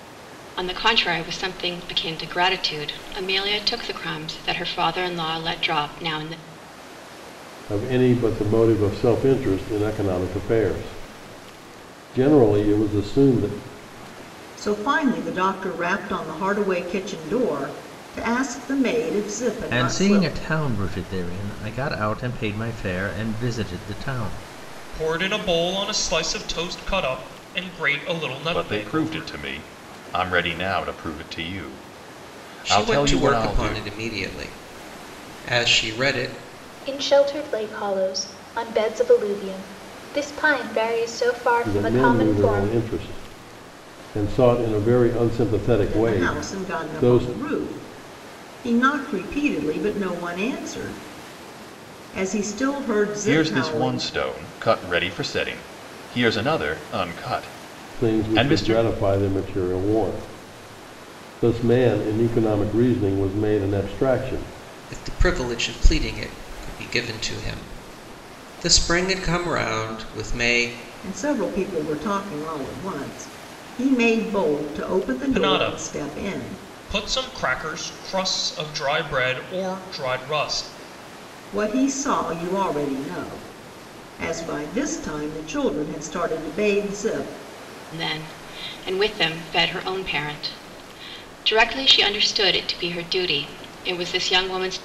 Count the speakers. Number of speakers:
eight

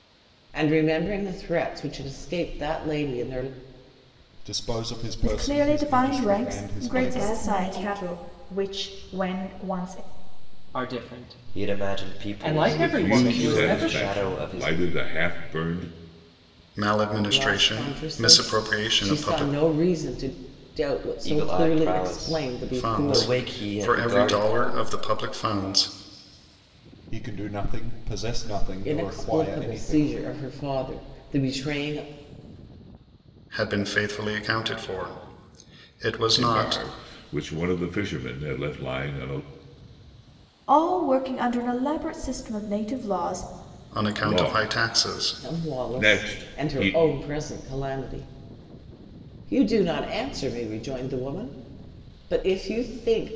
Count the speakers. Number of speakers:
eight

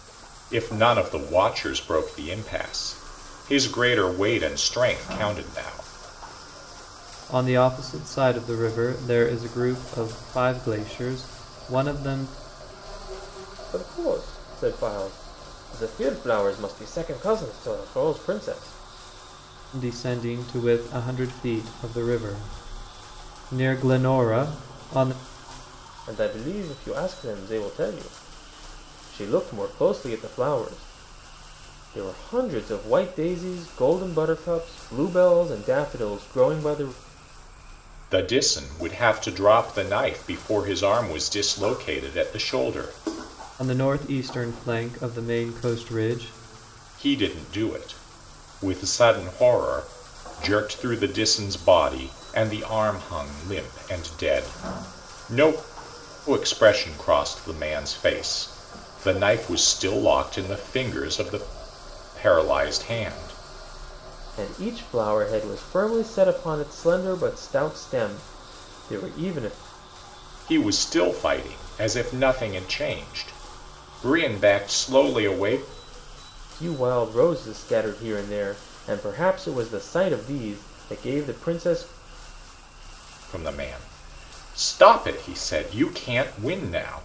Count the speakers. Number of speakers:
three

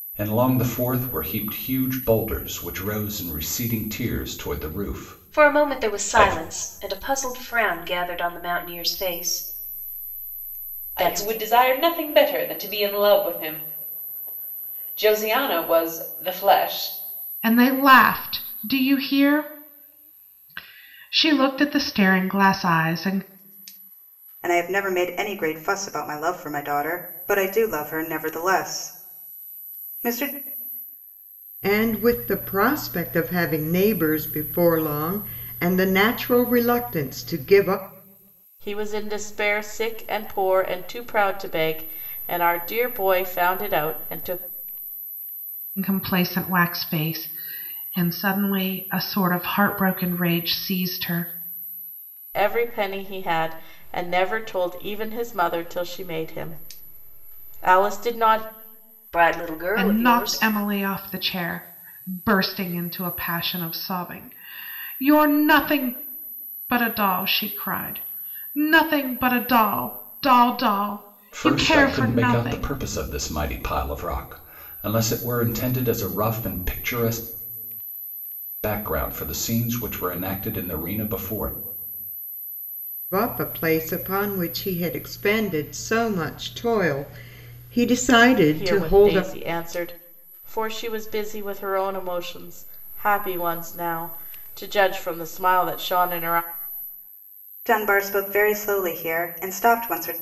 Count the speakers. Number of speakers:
seven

